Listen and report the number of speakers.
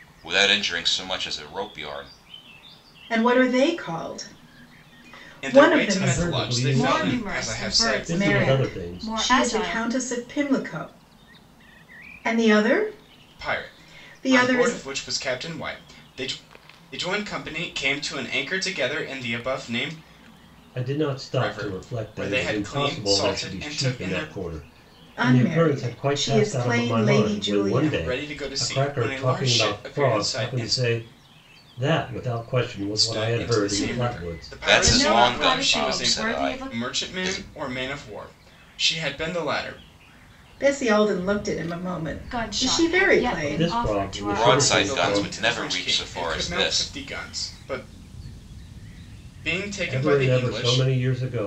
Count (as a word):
five